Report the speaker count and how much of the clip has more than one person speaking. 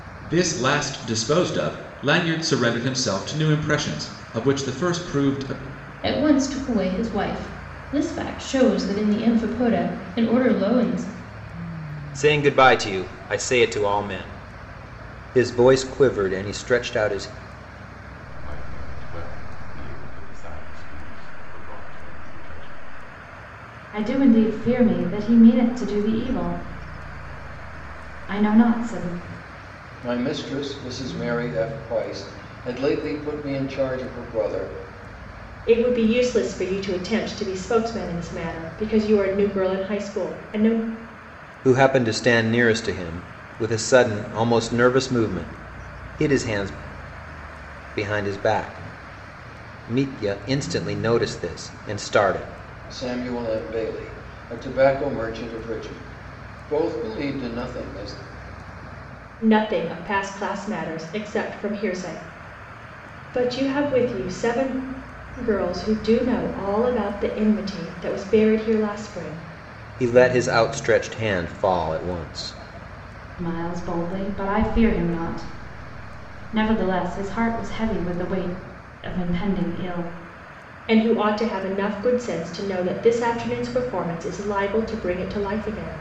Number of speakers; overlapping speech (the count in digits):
7, no overlap